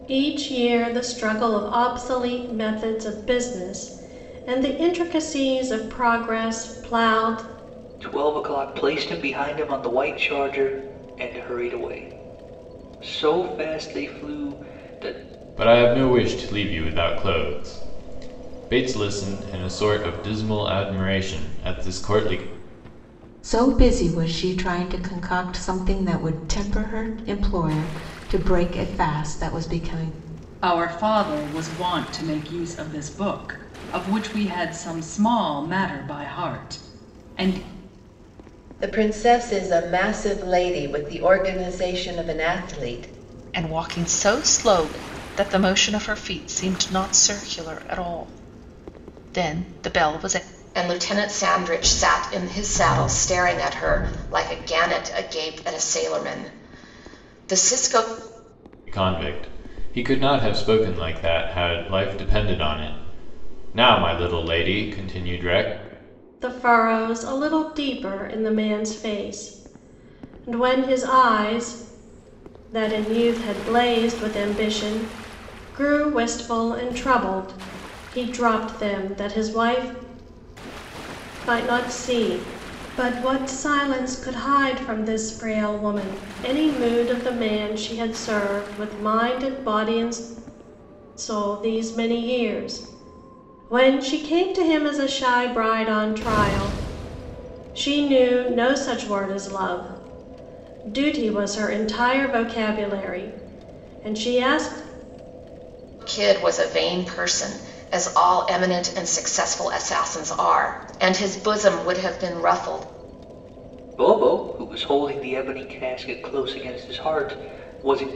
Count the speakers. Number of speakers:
8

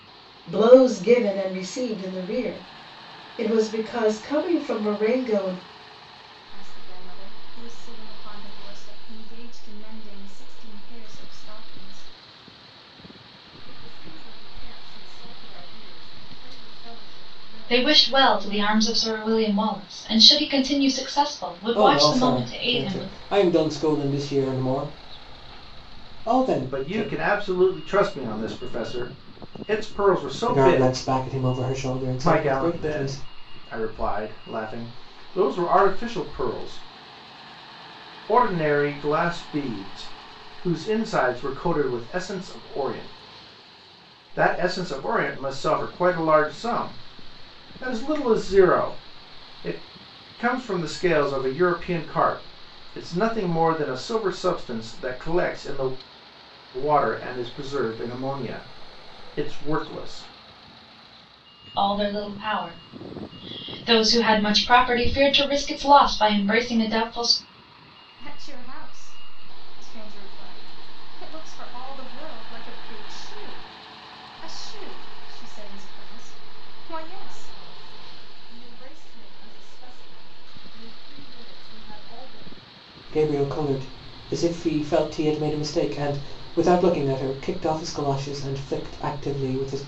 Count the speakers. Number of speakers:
6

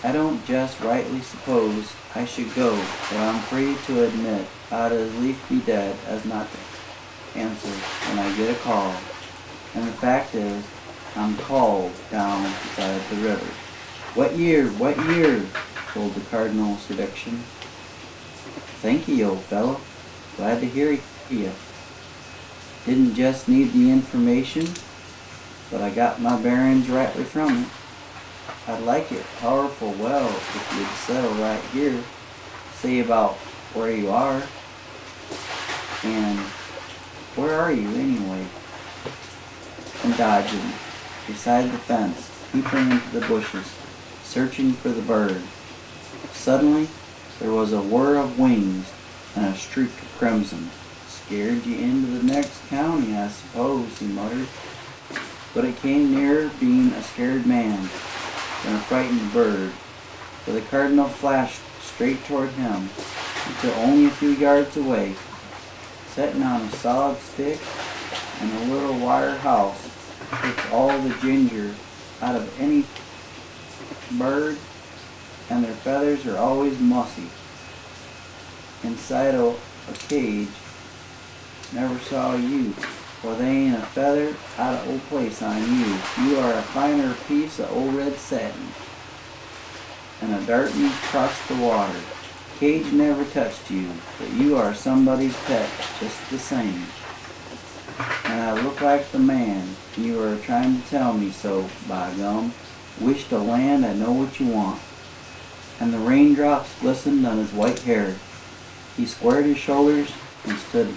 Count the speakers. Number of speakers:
1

